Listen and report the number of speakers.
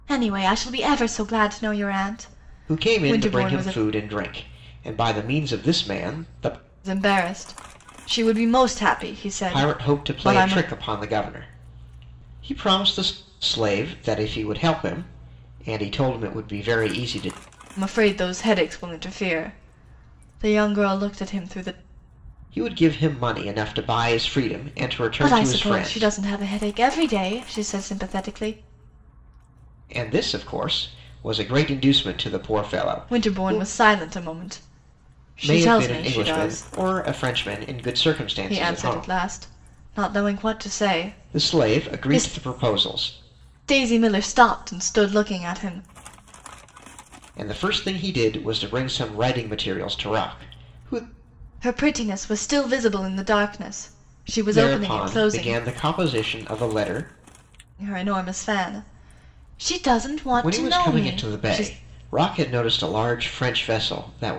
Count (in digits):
2